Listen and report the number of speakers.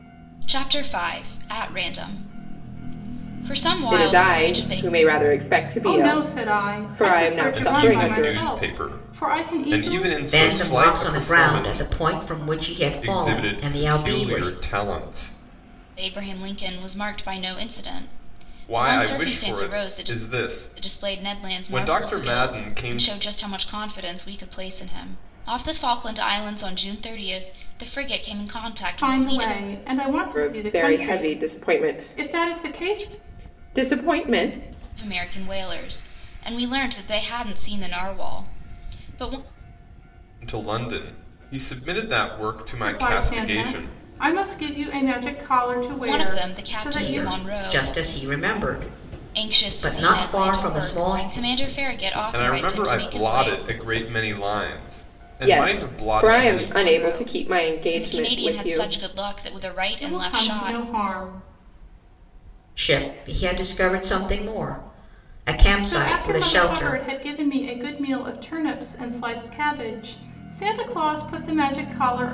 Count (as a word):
five